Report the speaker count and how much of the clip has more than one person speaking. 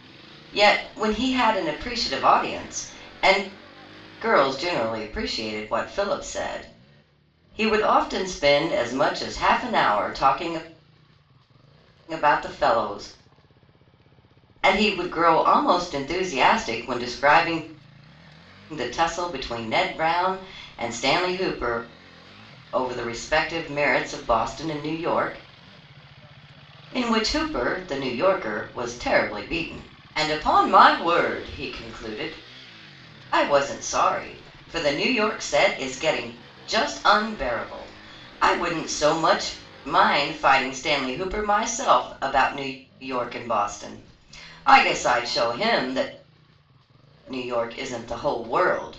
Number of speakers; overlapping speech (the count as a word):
one, no overlap